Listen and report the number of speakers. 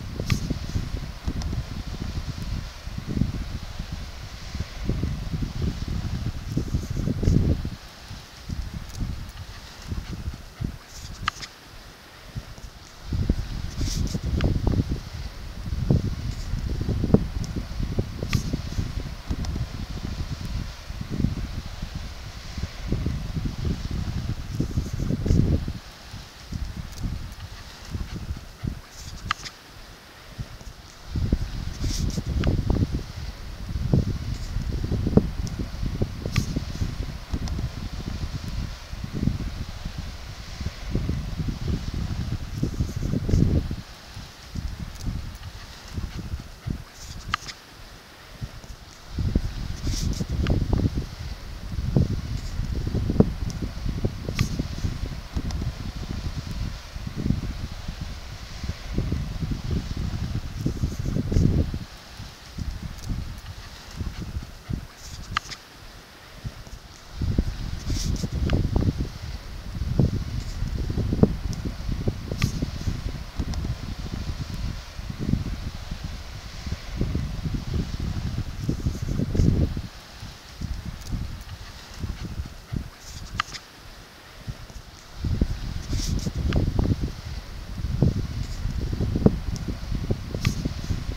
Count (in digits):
0